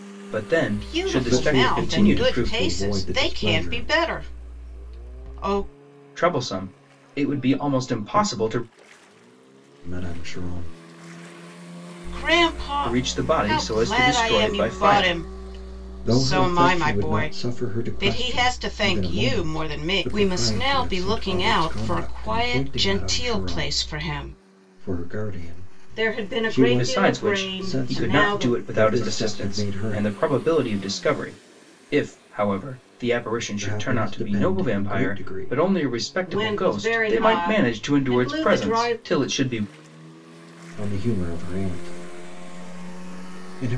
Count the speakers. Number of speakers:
3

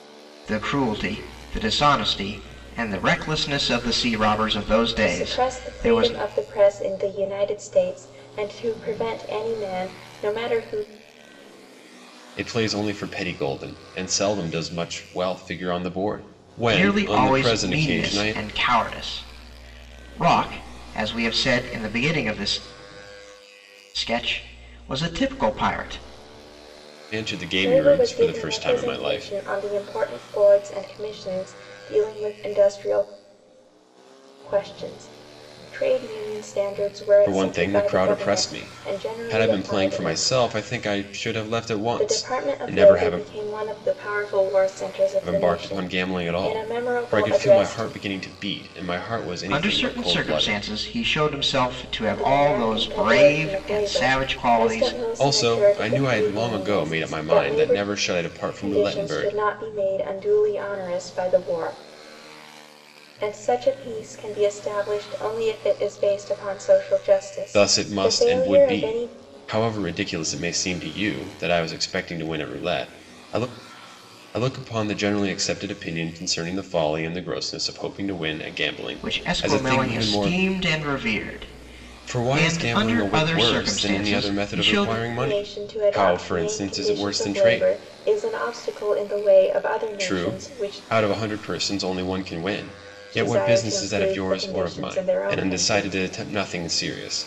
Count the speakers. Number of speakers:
3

